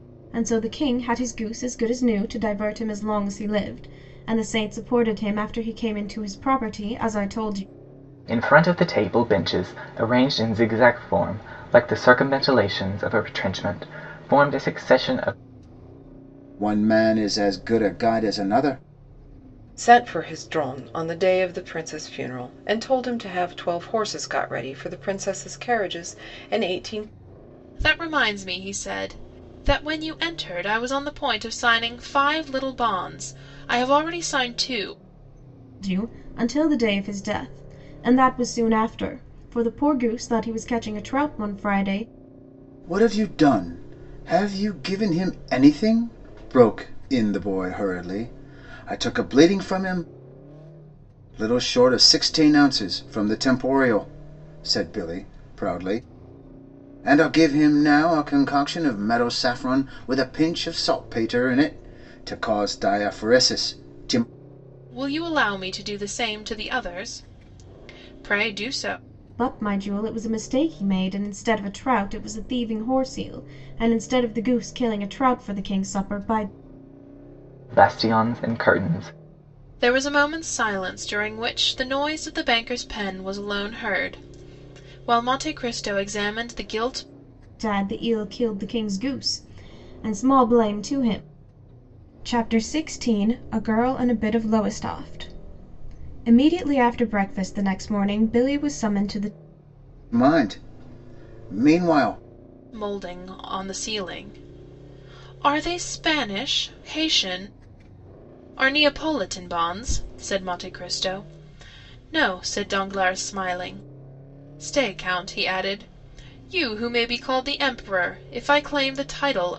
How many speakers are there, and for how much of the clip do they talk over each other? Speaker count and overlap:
five, no overlap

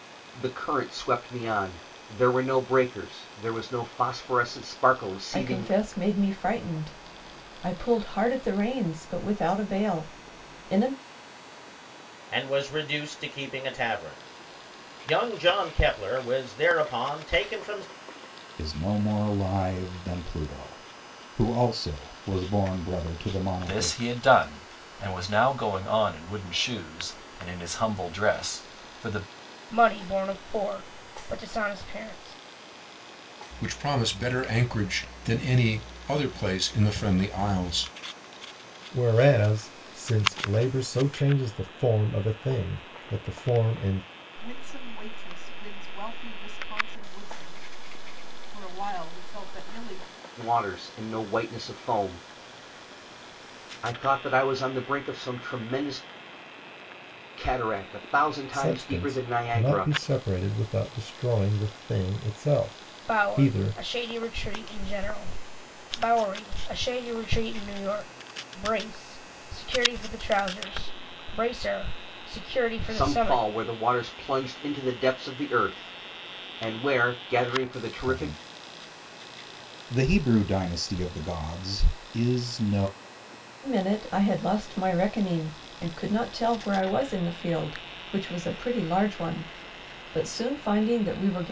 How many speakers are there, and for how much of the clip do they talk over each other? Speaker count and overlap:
nine, about 4%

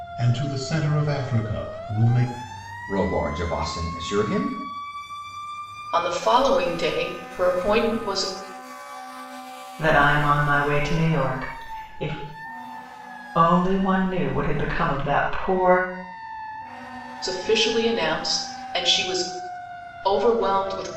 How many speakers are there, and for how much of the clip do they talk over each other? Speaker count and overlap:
four, no overlap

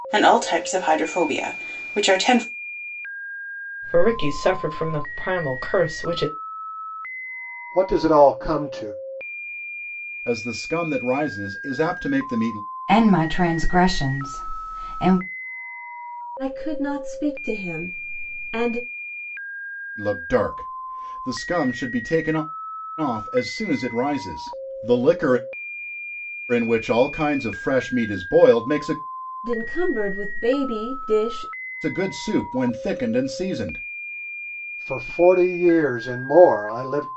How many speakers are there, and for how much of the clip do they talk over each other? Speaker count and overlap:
six, no overlap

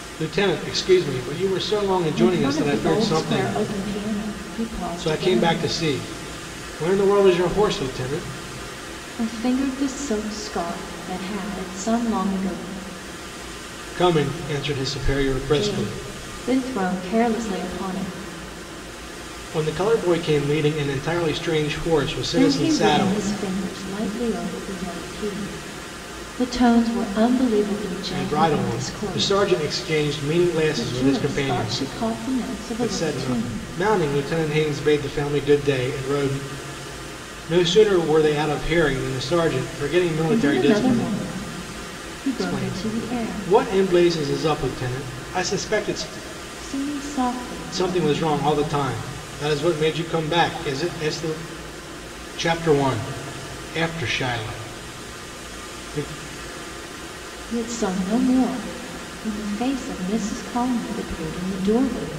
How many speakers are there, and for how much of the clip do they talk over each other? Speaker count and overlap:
two, about 16%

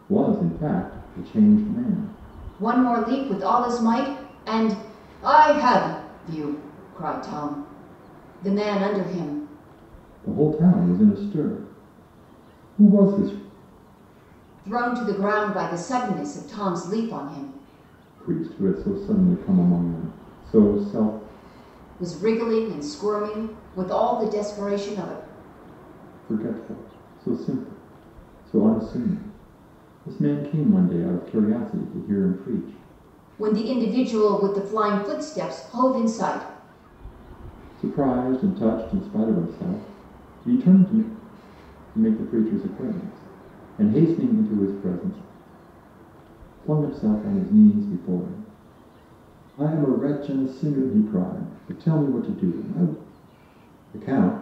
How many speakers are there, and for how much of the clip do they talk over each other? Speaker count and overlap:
two, no overlap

